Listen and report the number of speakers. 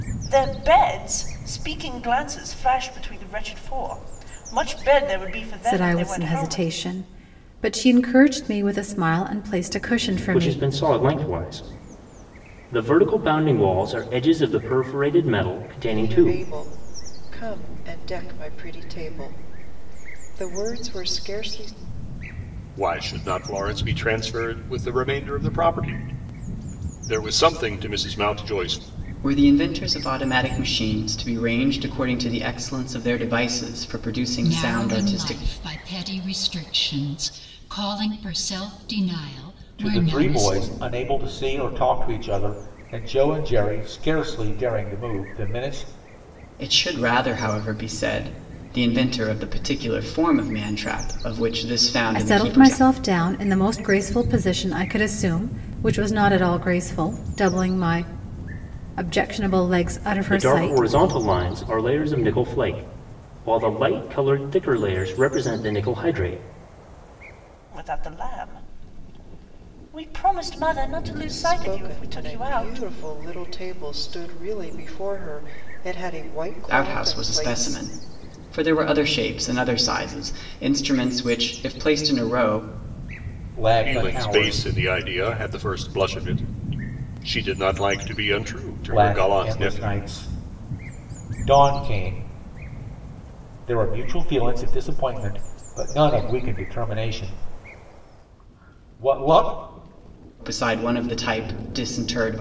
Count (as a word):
eight